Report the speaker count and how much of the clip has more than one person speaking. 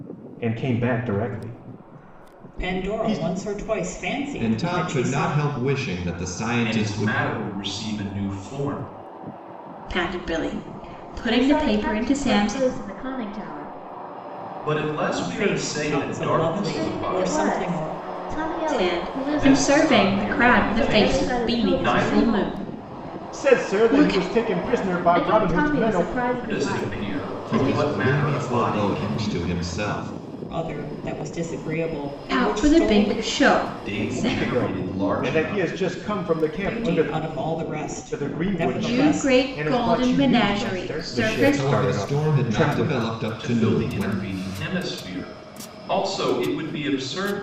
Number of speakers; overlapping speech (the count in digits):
6, about 52%